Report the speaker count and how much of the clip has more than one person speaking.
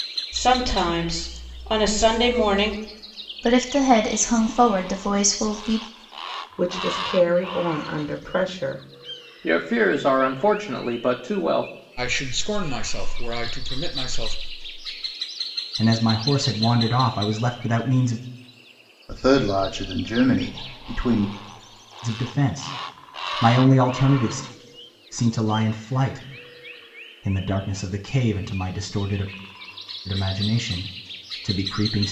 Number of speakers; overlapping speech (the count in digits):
7, no overlap